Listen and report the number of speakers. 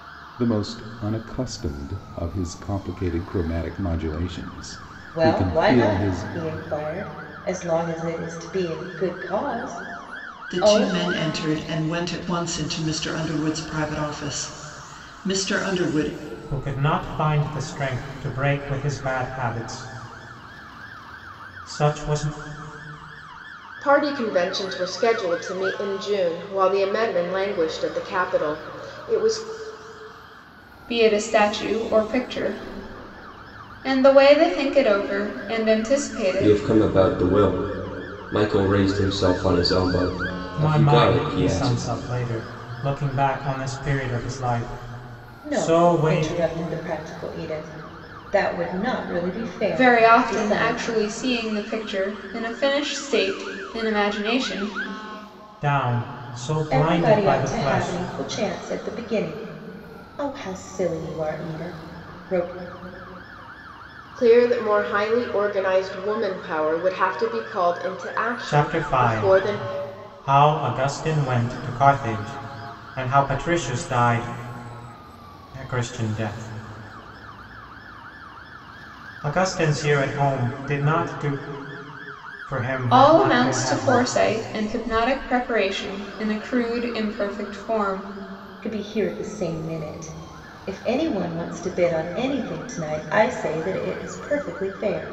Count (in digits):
7